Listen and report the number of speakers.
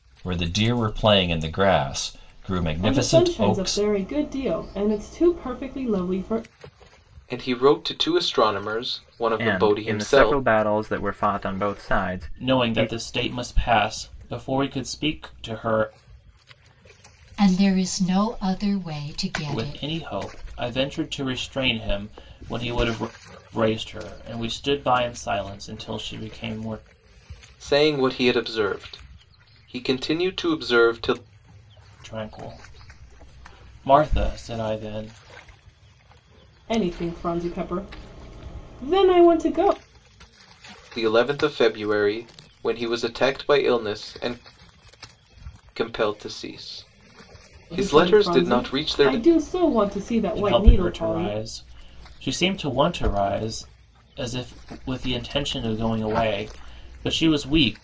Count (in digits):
6